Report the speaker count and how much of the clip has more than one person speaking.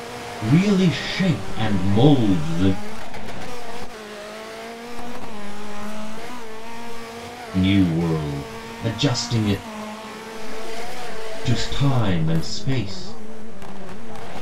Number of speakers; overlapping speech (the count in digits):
2, about 22%